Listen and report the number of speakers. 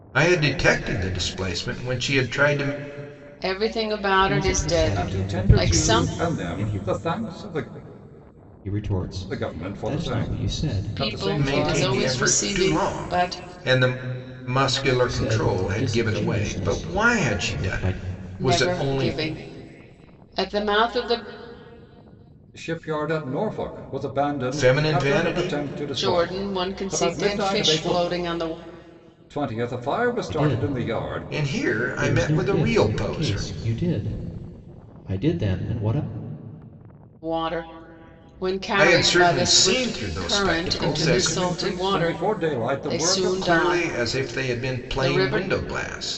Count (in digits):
4